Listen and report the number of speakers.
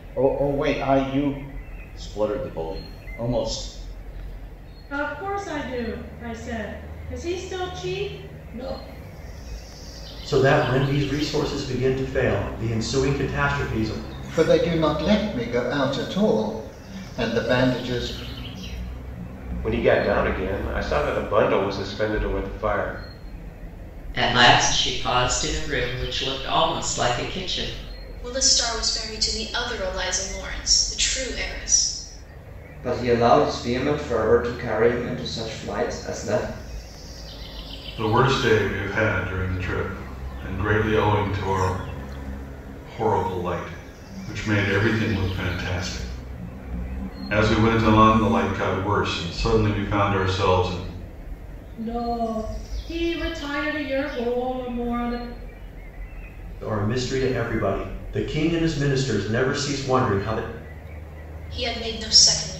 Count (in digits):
9